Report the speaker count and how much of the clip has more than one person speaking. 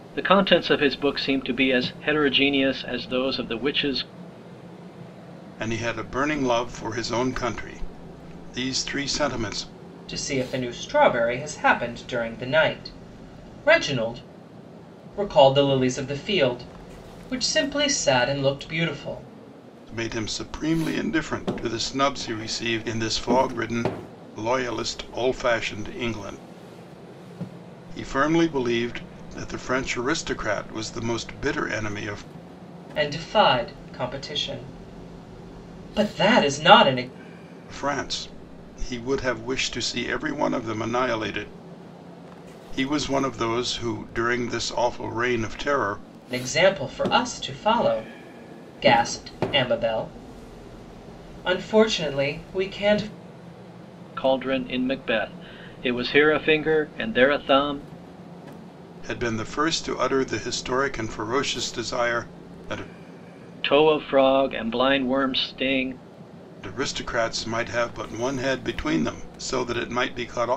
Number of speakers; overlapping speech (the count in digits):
3, no overlap